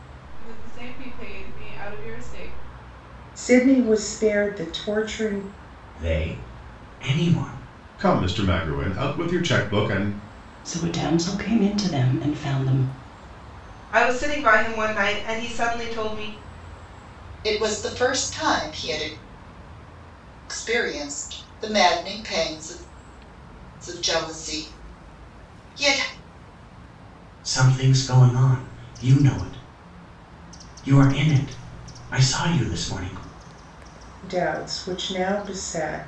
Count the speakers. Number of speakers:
7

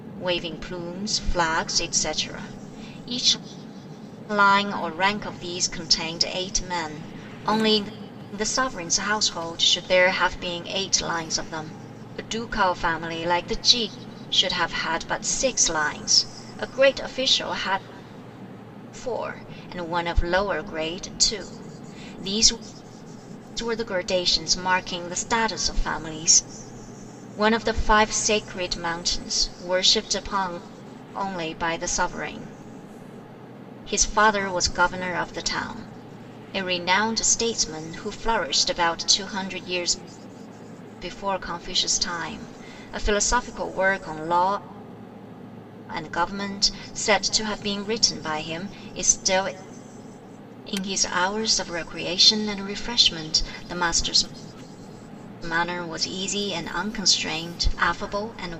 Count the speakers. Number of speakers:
1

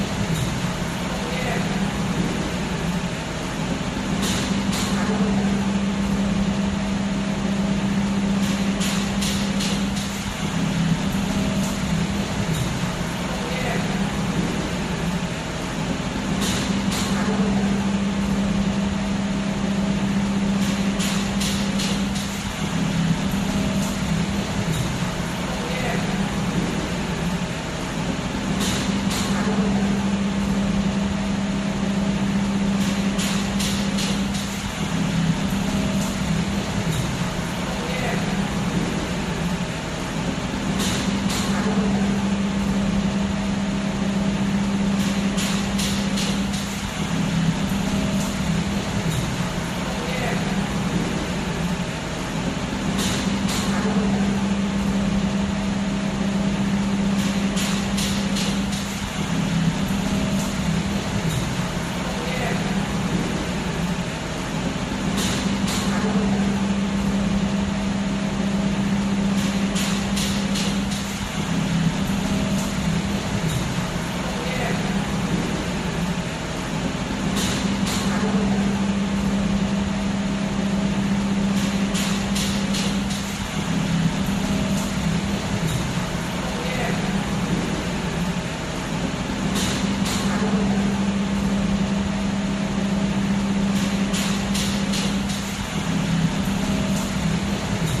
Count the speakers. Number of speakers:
0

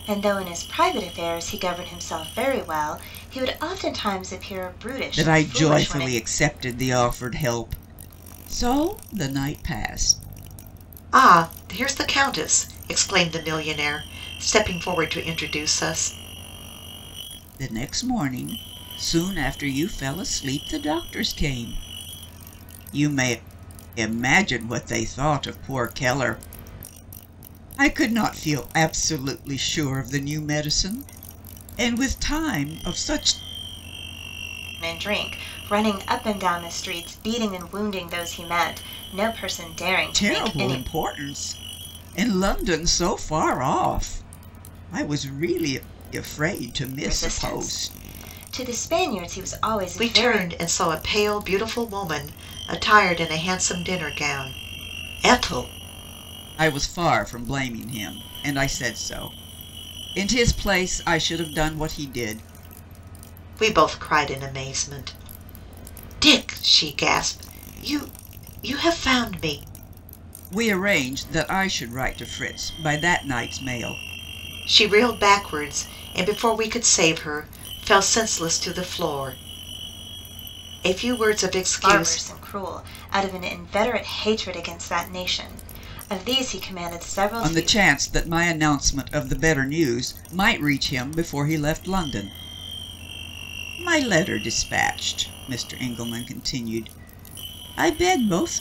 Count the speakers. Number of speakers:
3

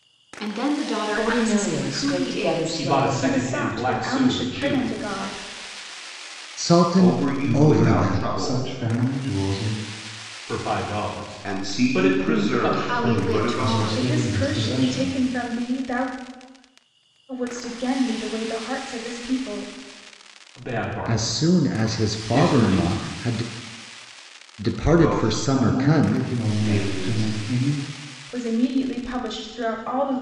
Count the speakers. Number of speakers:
7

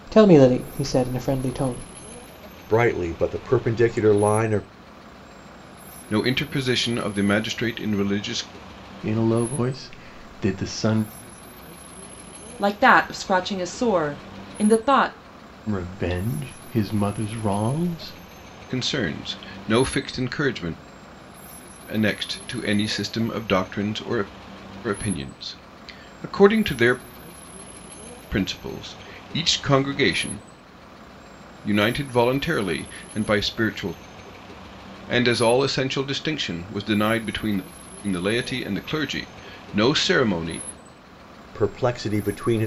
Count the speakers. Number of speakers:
5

